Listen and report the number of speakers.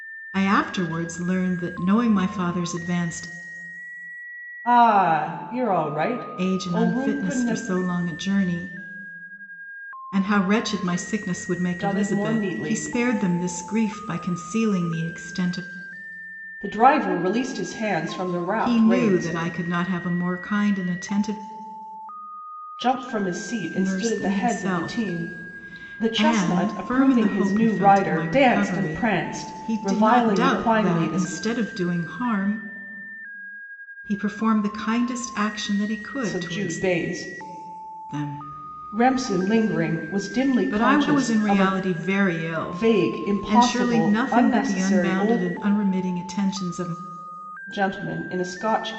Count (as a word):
two